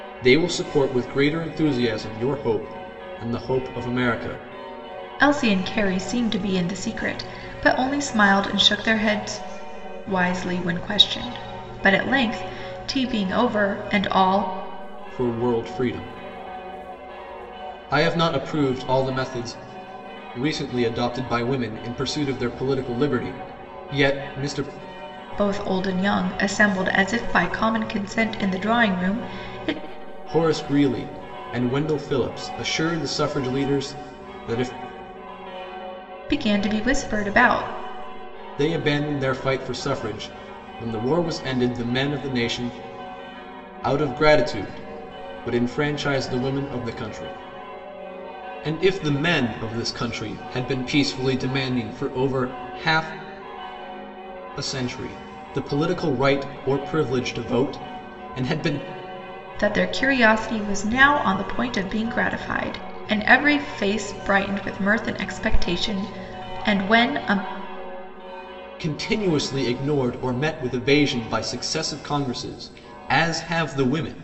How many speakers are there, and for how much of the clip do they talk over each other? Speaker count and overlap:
2, no overlap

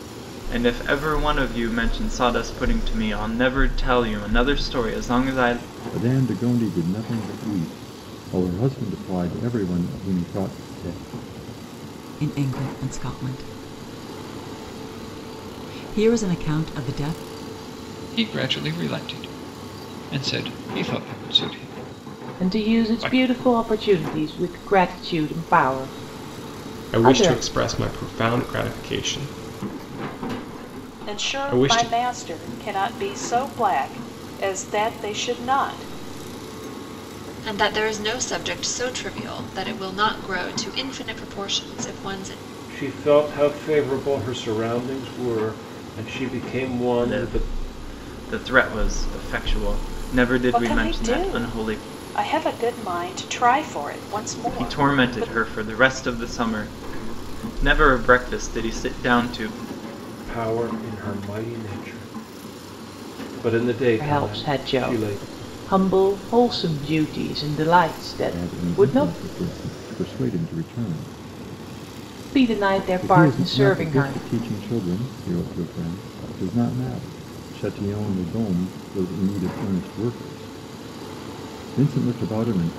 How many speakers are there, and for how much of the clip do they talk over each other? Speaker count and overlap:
9, about 11%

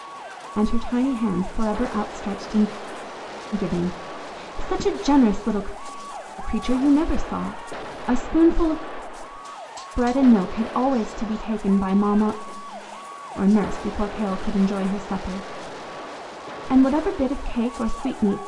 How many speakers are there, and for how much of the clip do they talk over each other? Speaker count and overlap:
1, no overlap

